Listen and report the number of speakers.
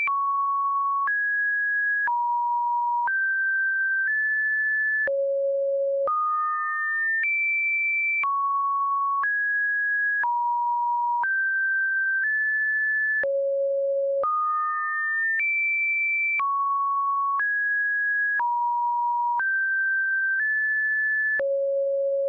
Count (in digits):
0